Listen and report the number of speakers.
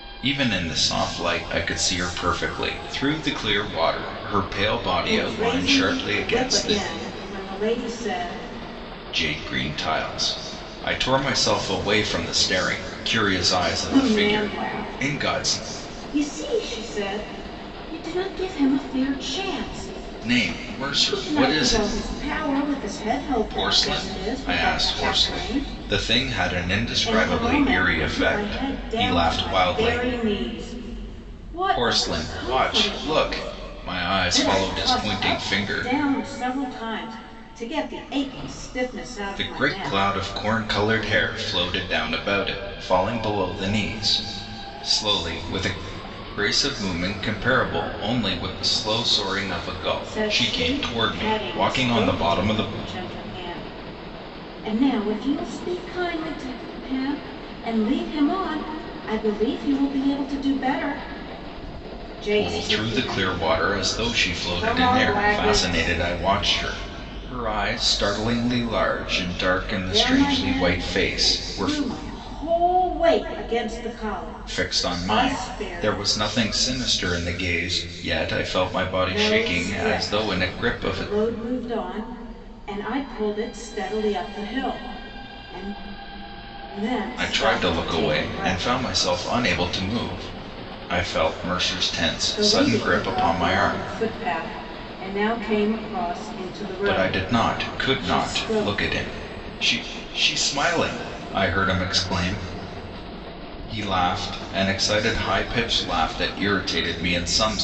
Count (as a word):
two